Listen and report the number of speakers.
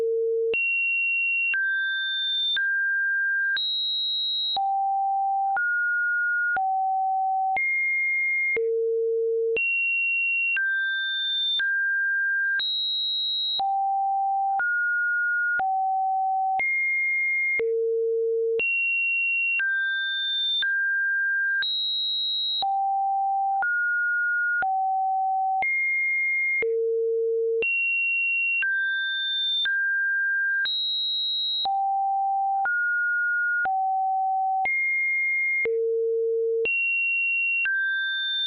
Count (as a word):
zero